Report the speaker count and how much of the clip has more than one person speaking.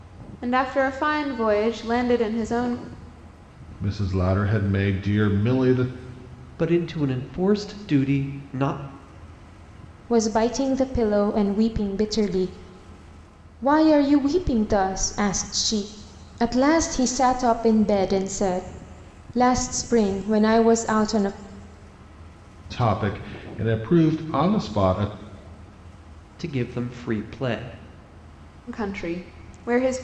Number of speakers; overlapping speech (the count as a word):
four, no overlap